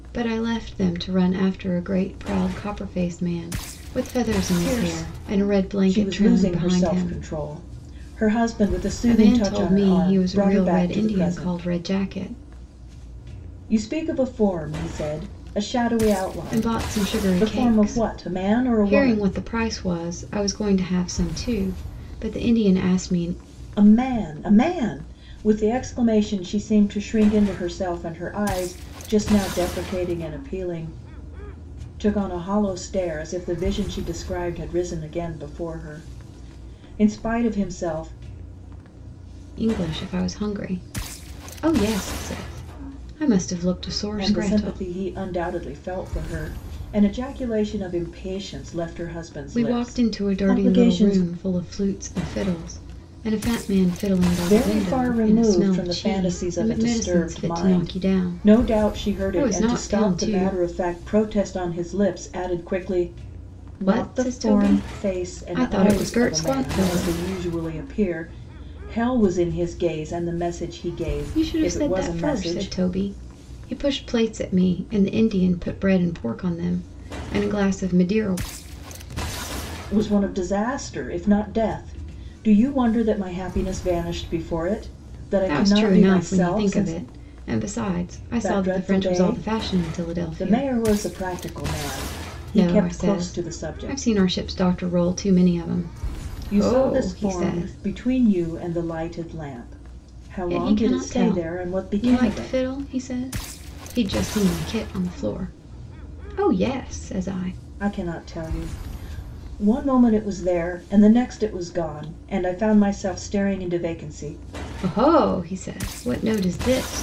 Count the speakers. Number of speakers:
2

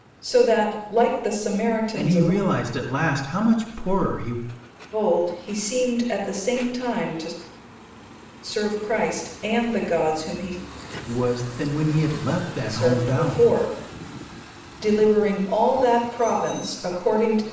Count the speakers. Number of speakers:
2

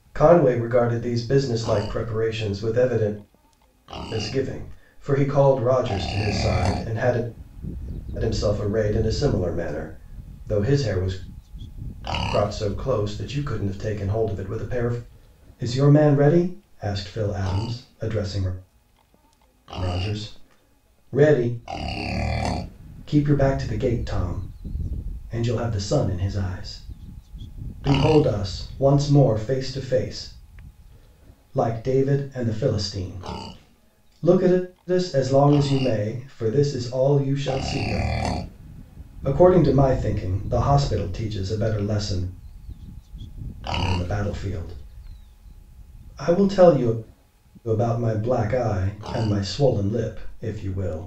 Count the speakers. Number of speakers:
1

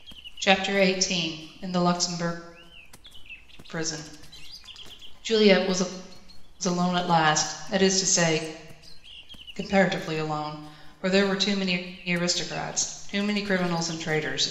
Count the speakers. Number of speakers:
1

